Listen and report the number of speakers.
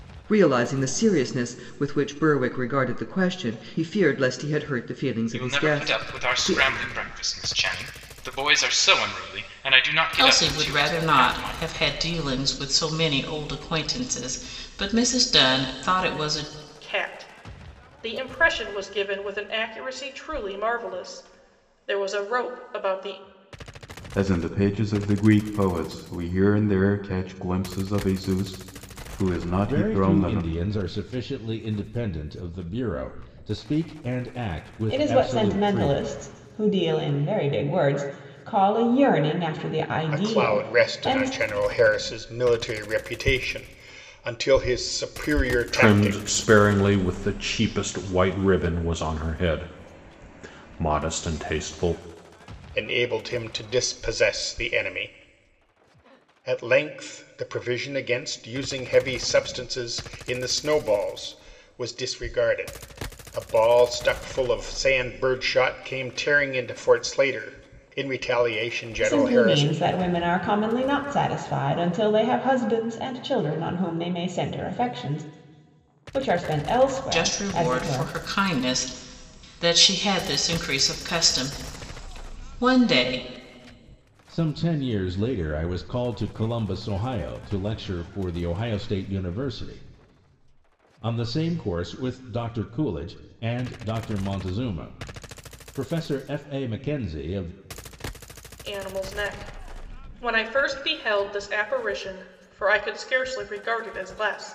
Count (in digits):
9